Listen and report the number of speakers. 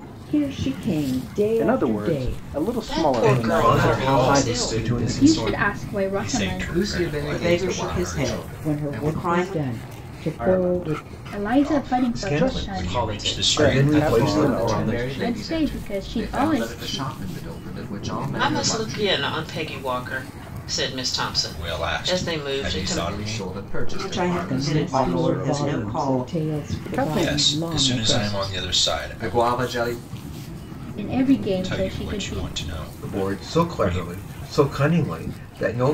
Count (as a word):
nine